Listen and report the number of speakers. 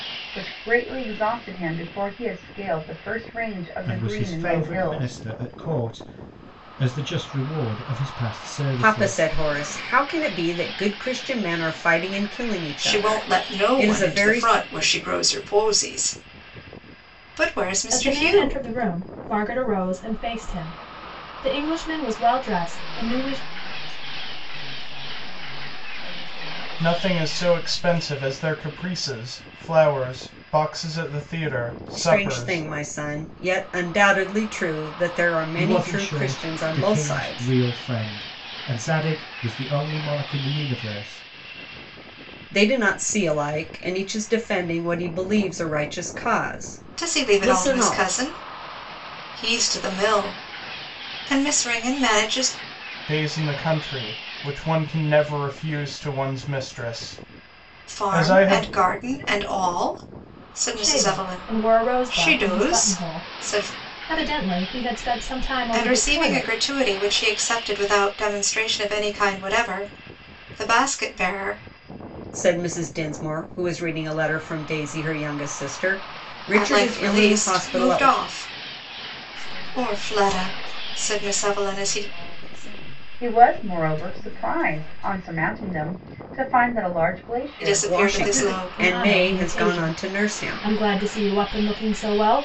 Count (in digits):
7